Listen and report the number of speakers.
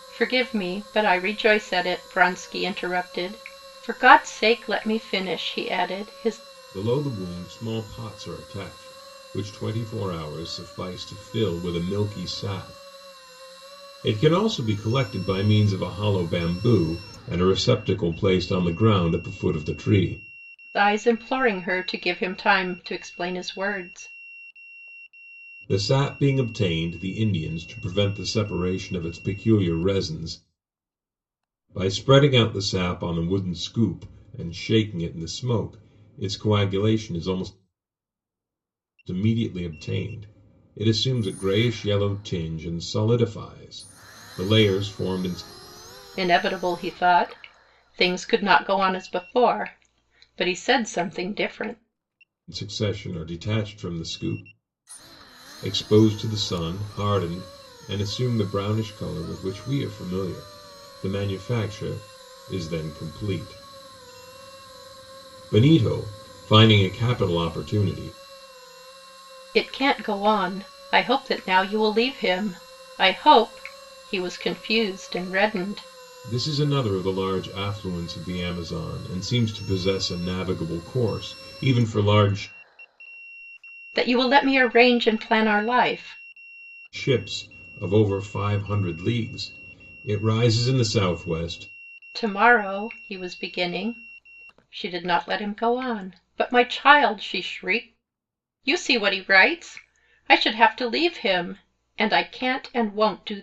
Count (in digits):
2